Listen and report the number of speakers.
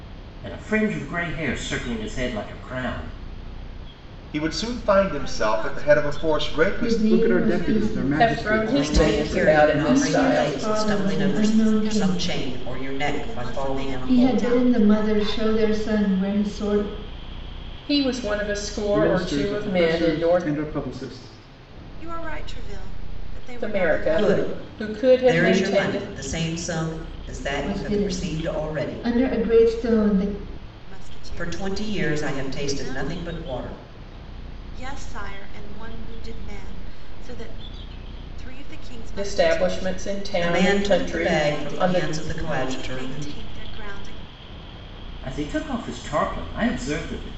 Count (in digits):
7